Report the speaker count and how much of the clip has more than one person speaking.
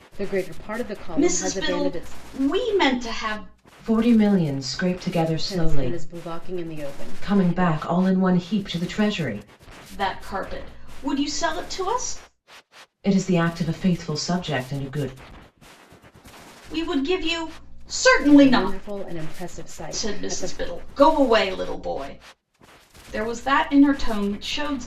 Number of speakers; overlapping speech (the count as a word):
three, about 14%